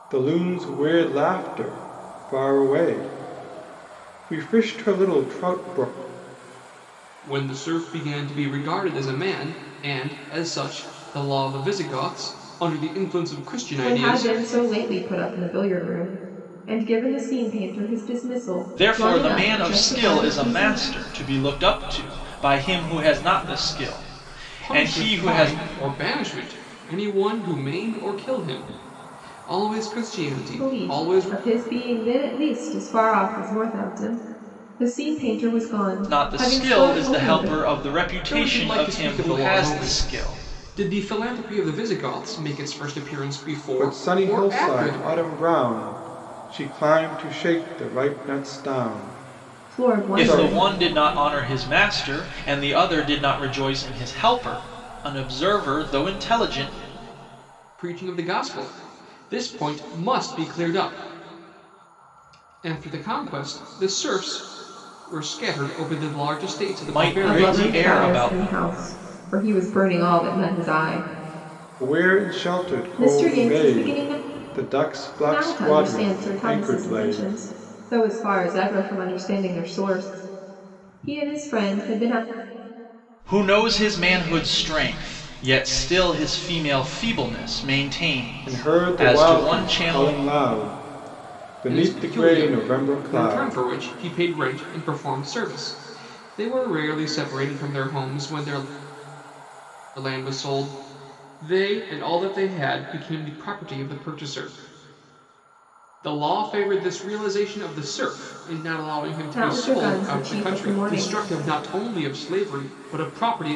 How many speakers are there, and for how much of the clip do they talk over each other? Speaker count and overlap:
four, about 20%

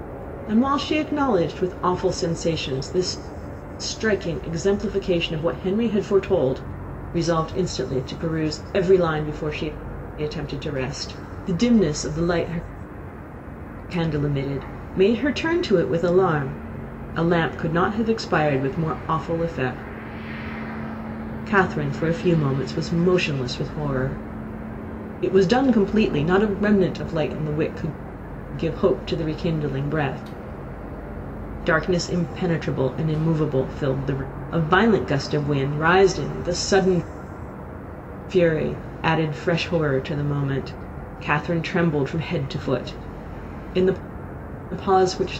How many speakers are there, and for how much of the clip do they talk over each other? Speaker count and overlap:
one, no overlap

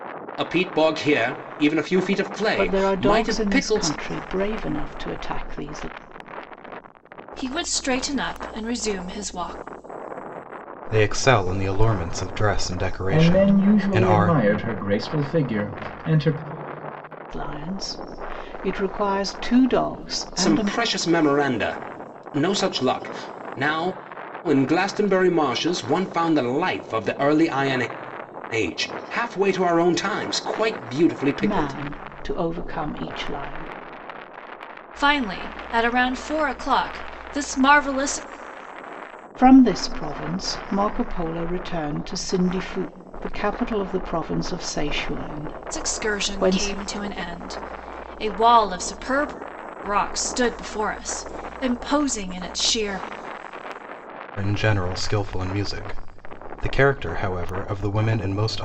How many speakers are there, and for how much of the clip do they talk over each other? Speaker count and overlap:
five, about 8%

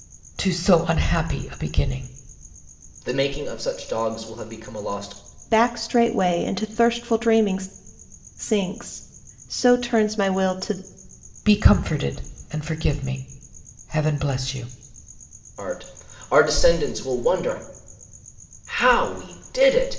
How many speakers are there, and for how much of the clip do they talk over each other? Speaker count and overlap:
three, no overlap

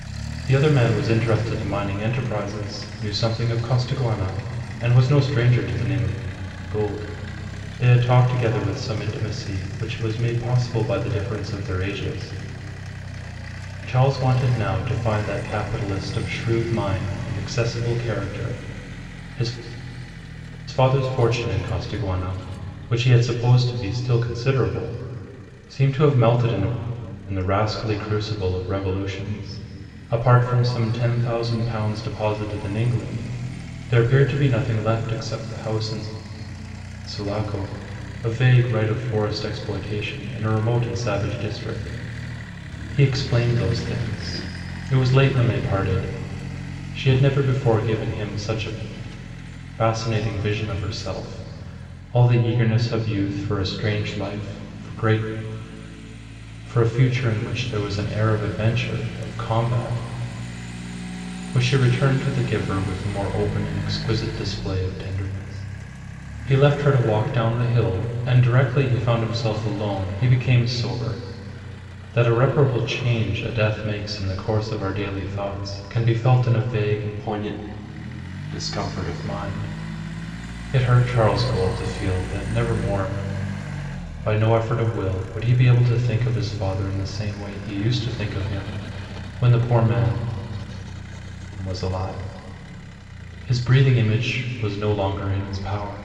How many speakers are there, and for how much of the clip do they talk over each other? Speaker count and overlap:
one, no overlap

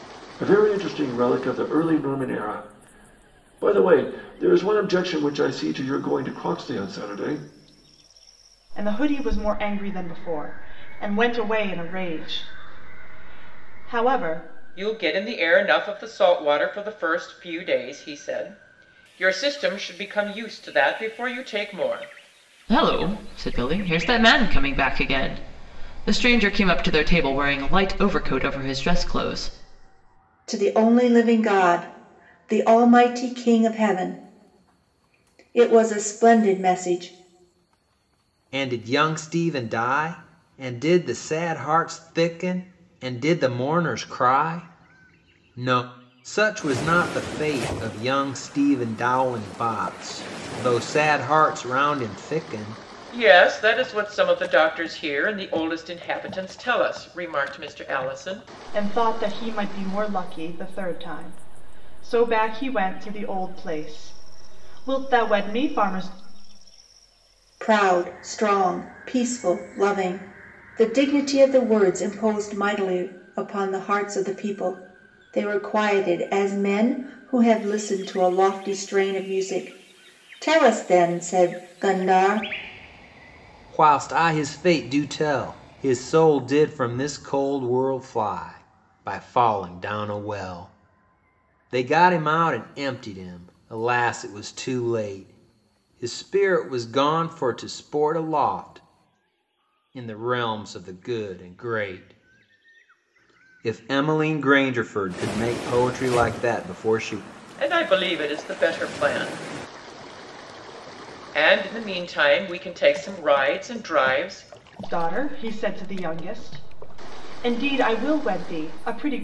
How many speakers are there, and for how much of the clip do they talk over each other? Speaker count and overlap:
six, no overlap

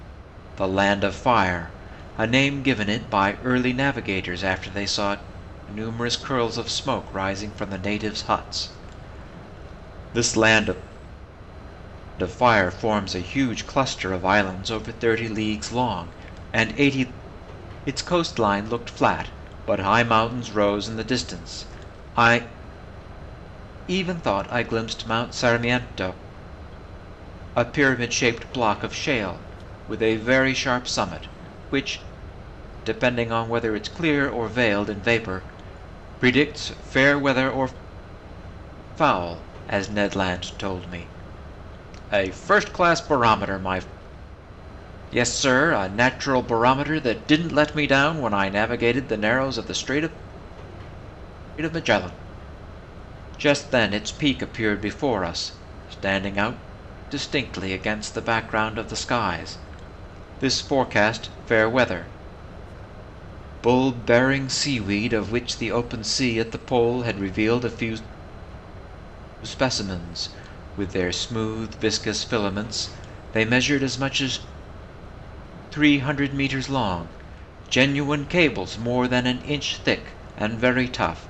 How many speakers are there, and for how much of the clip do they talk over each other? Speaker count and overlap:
one, no overlap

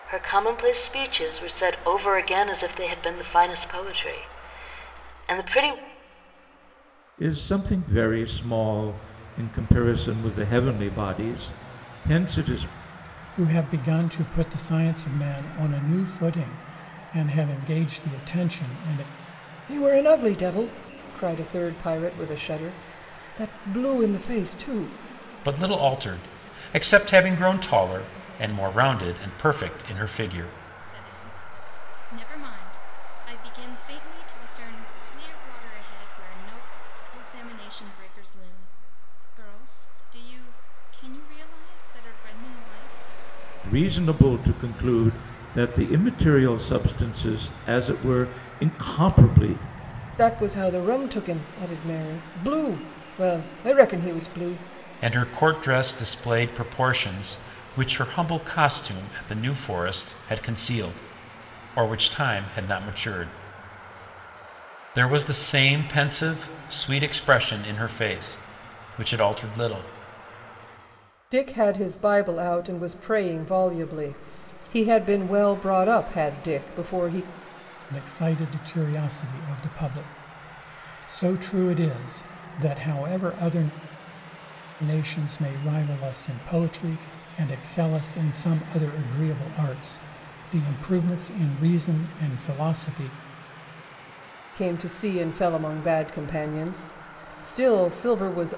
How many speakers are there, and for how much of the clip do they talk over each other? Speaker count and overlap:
six, no overlap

